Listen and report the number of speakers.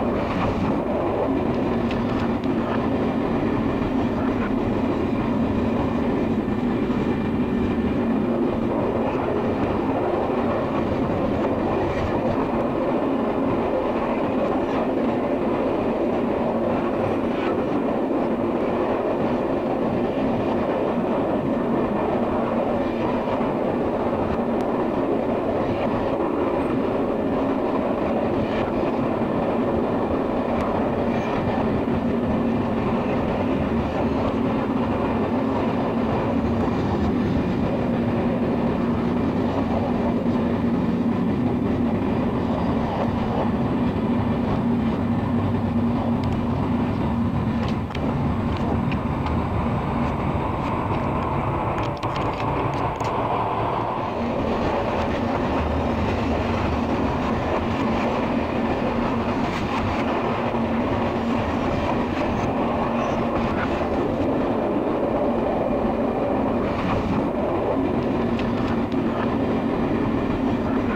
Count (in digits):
0